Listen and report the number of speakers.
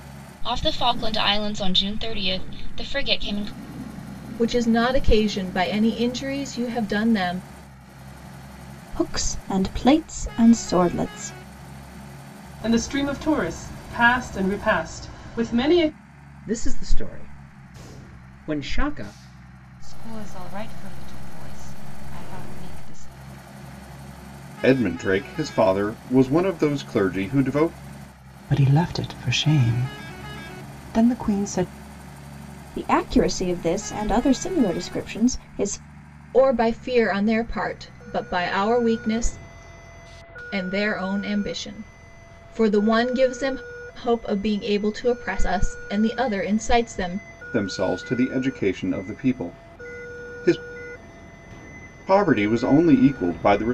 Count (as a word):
eight